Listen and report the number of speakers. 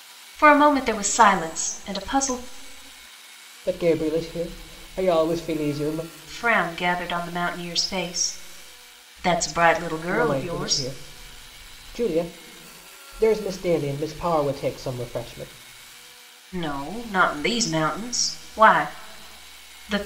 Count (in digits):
2